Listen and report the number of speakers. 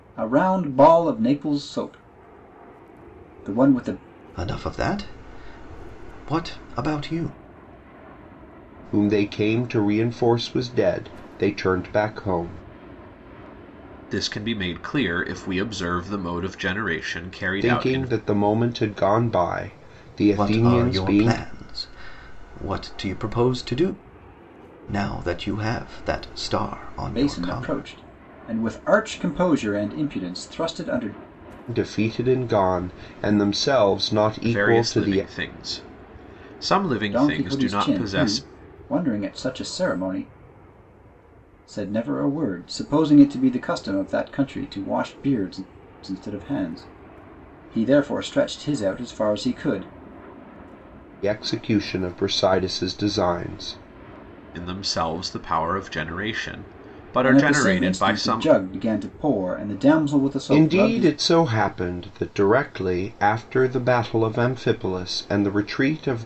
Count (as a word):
four